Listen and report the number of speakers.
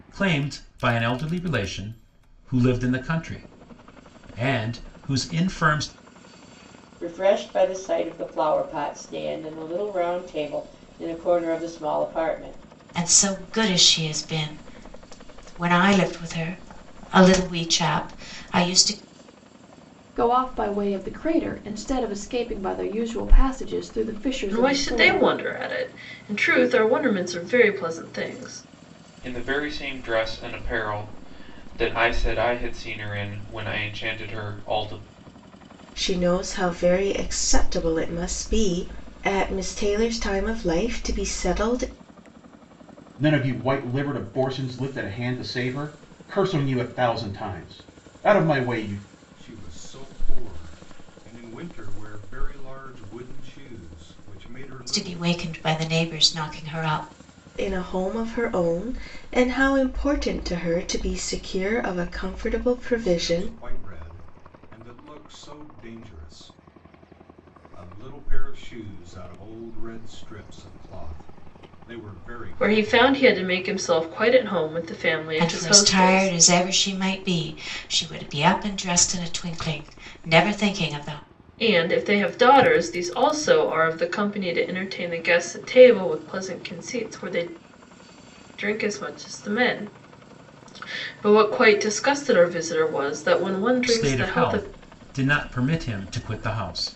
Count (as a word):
nine